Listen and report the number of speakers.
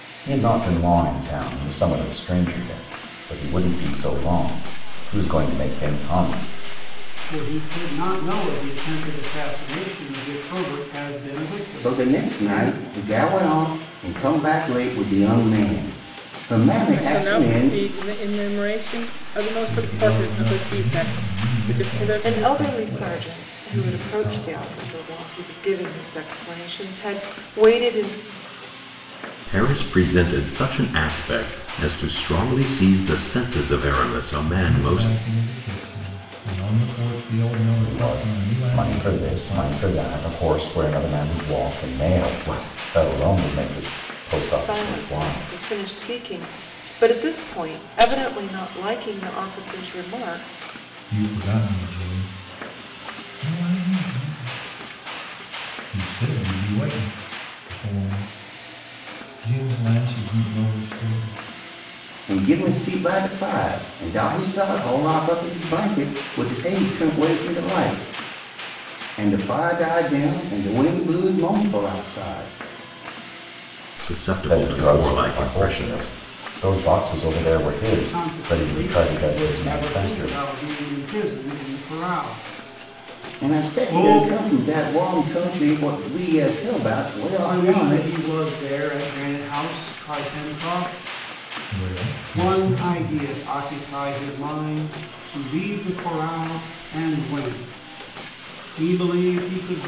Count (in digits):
8